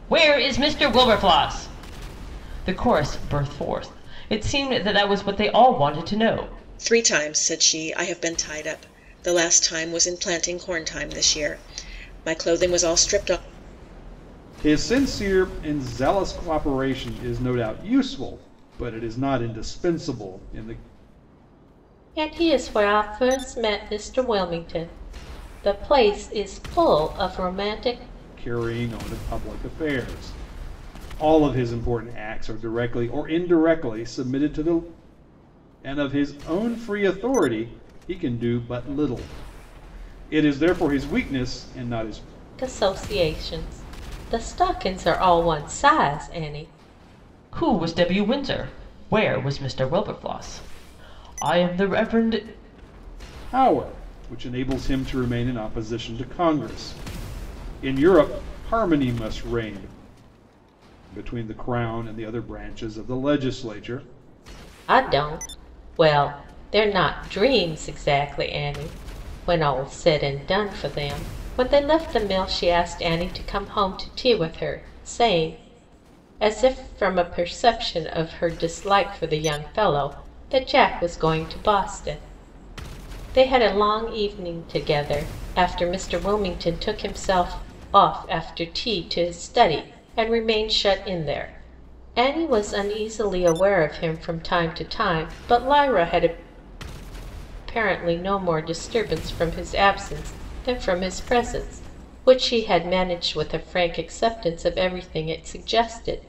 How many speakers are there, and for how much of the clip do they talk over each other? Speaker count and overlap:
4, no overlap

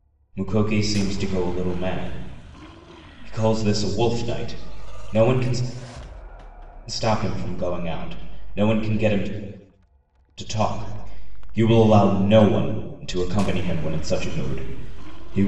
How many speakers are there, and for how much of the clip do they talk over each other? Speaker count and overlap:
1, no overlap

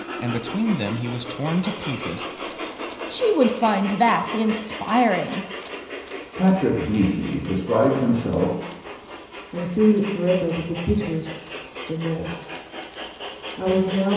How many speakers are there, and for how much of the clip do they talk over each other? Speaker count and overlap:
4, no overlap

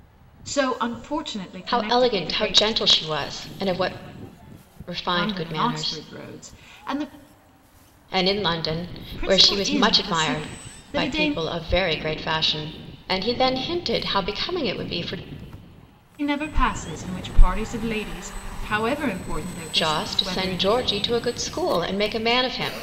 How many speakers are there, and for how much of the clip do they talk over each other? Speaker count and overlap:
2, about 22%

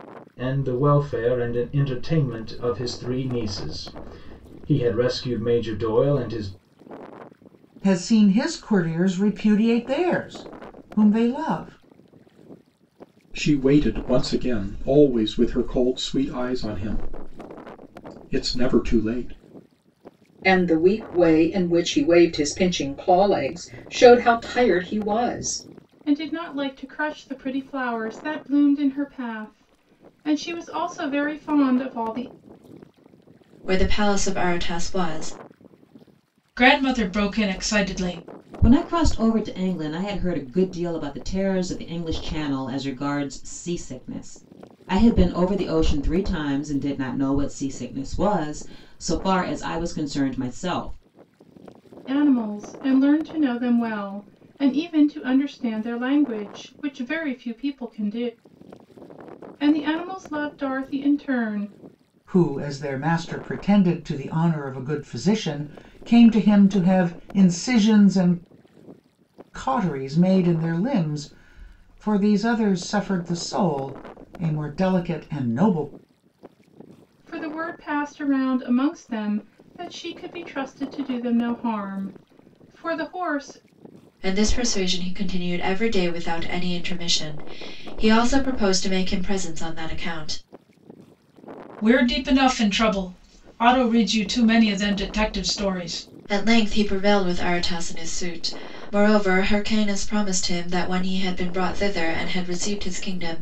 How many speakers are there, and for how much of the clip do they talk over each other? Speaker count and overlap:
8, no overlap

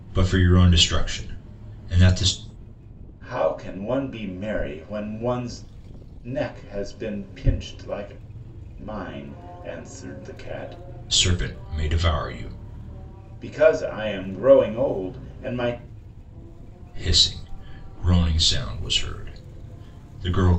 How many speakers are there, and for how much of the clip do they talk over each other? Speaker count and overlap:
2, no overlap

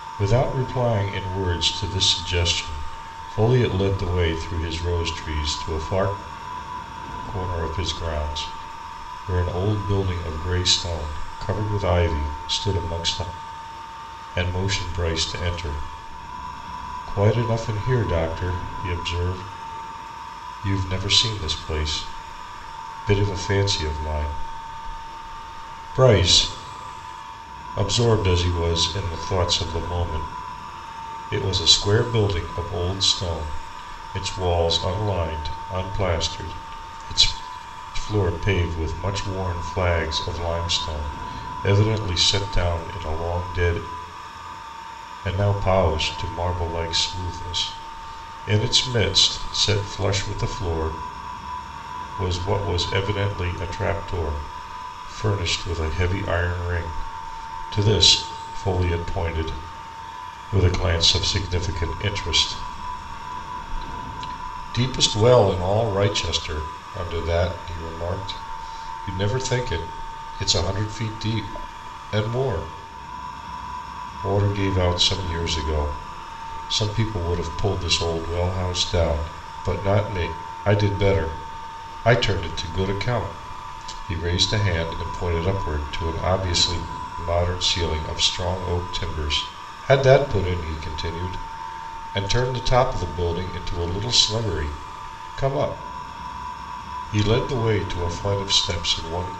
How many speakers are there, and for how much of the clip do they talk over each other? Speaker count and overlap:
1, no overlap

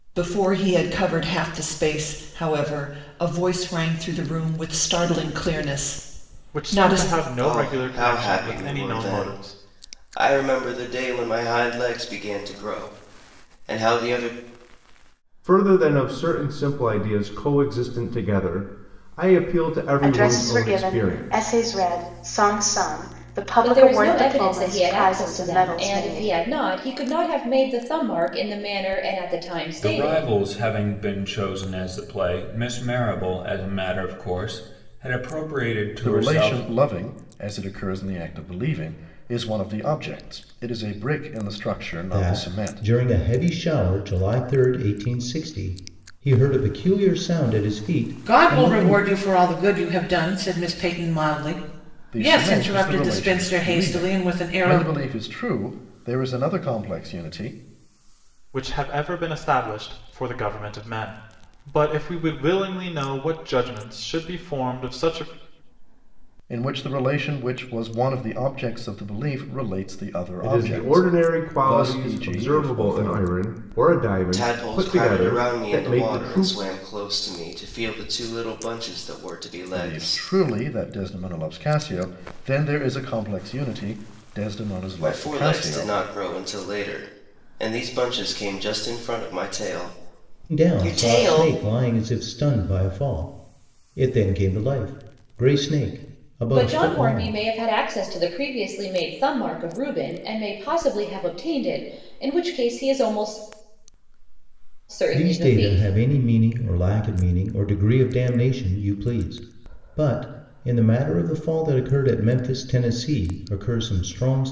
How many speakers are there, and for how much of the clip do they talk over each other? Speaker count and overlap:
10, about 19%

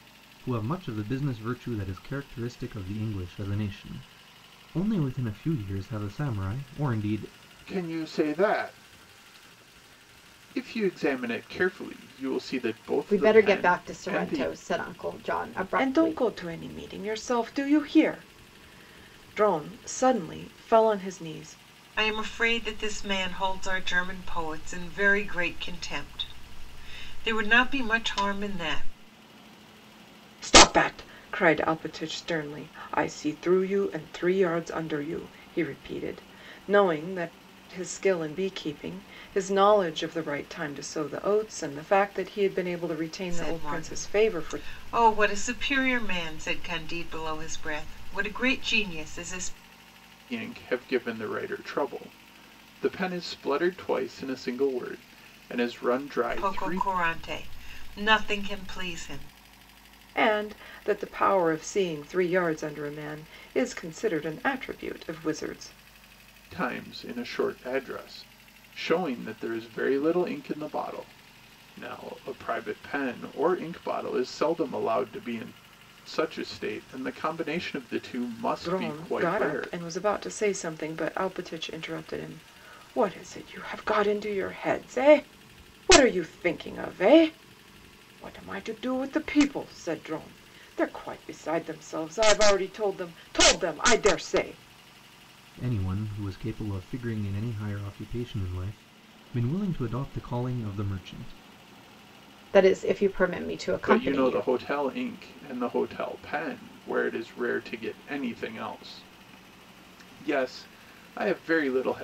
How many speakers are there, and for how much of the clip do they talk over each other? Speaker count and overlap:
5, about 5%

